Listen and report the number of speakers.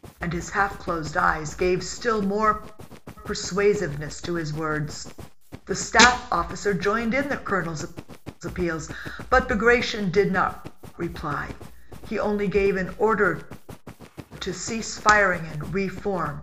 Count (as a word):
one